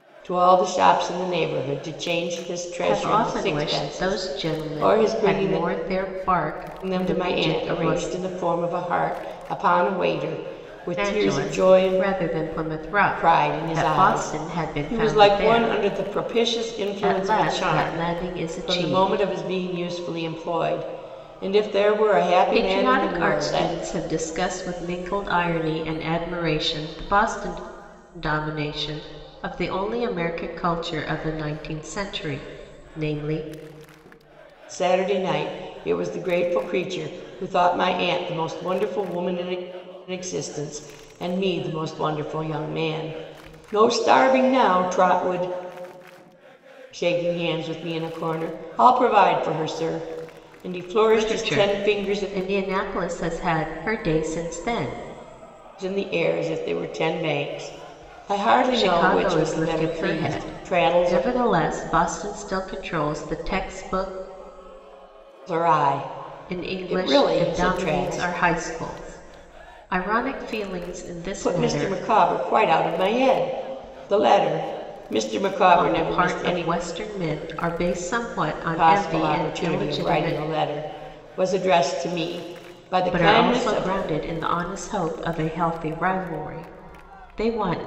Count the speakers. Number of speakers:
two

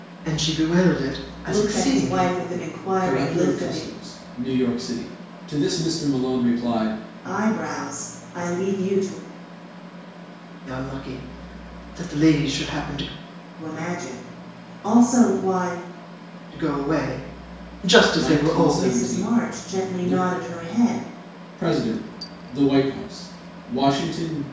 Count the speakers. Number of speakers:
three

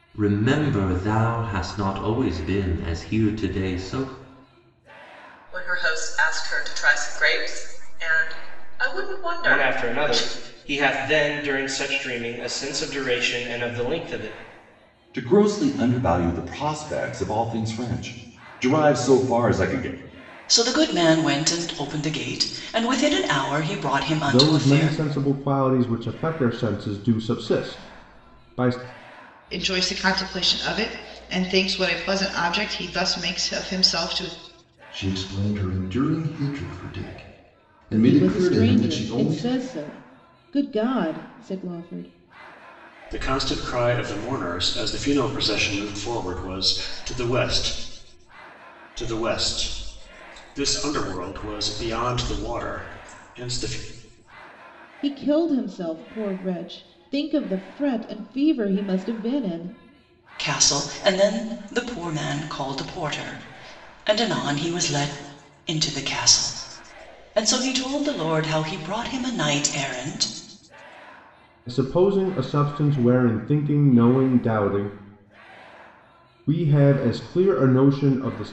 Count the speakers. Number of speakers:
ten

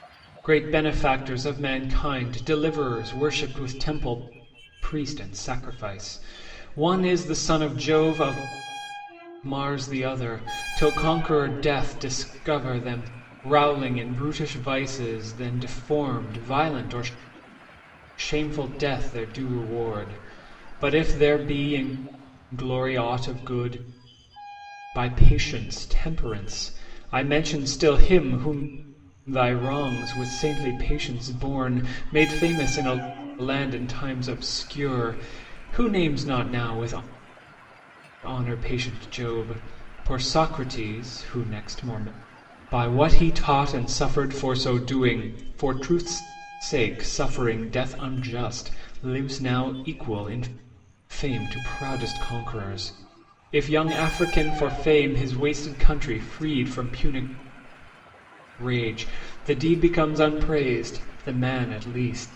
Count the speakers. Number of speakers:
one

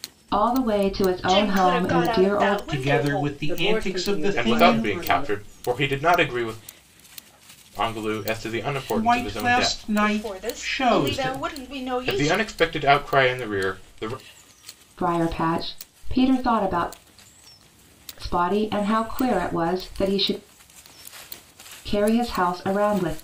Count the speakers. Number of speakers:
five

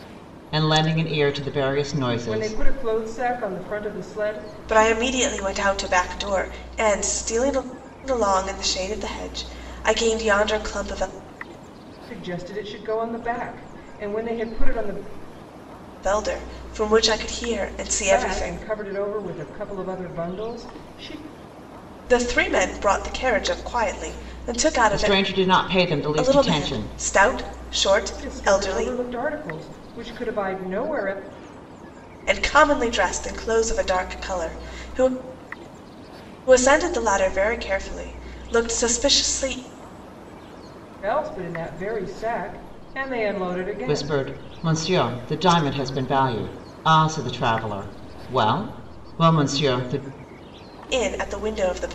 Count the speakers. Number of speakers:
three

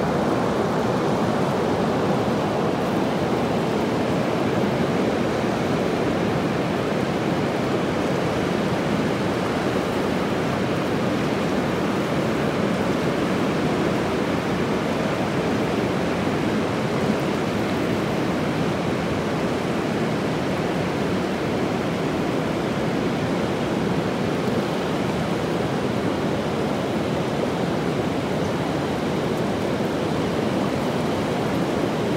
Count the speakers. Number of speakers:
zero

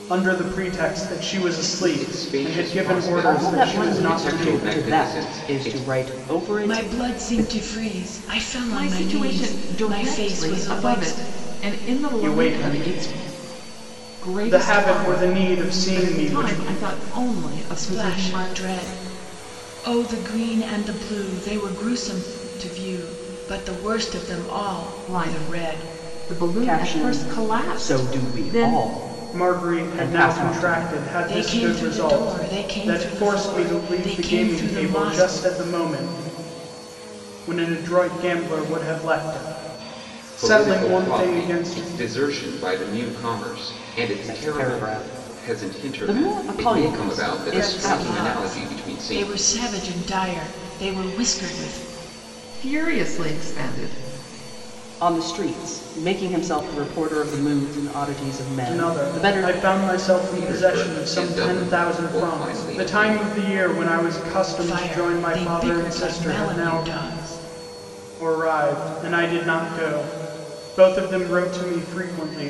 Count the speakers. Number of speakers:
five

